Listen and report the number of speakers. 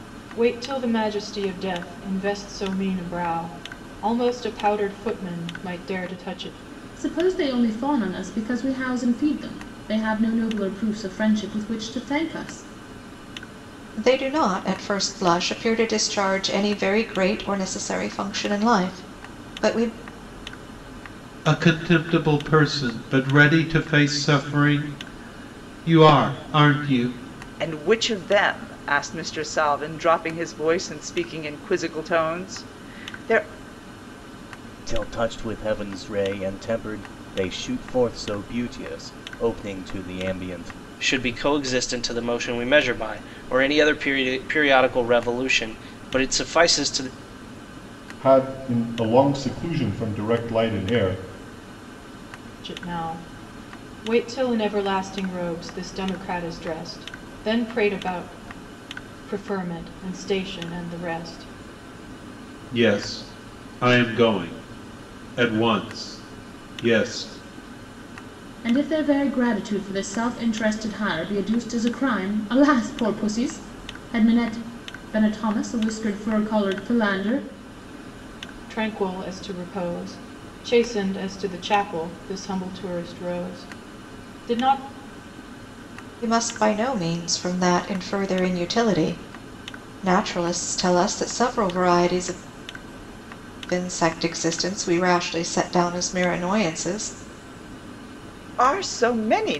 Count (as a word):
eight